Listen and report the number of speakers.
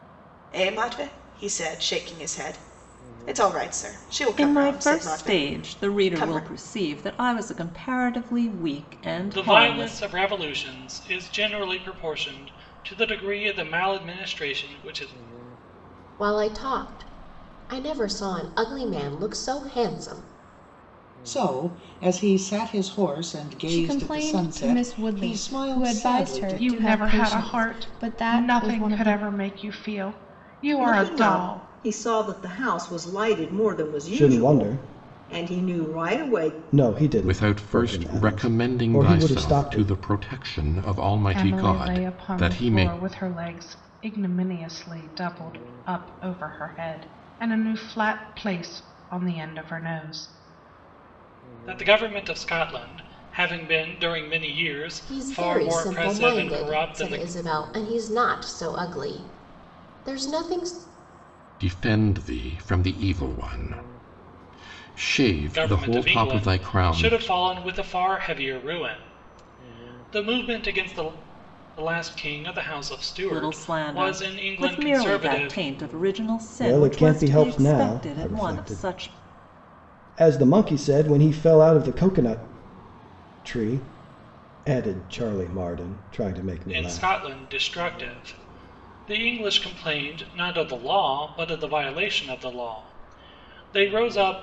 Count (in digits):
10